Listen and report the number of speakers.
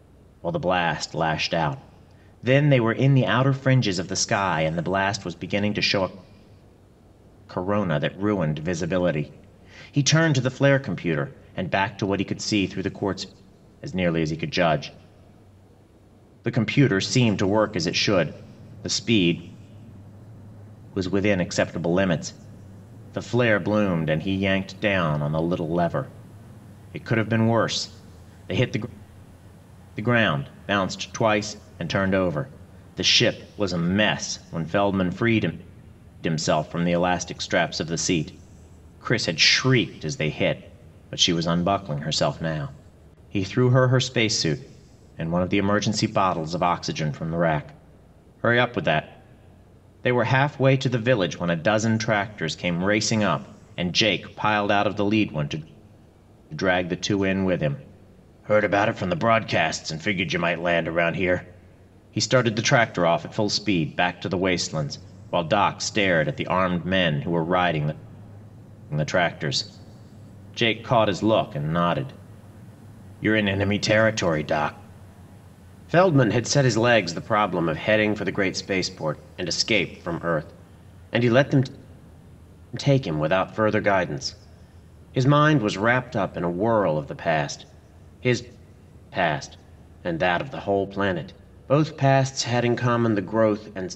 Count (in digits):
1